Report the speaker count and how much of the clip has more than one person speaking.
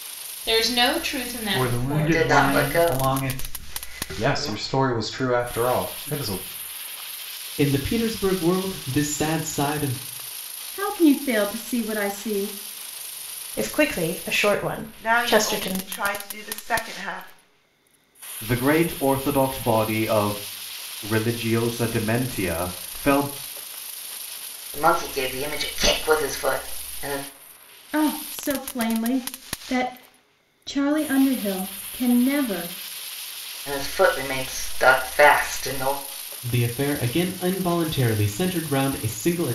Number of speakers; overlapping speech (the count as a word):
nine, about 9%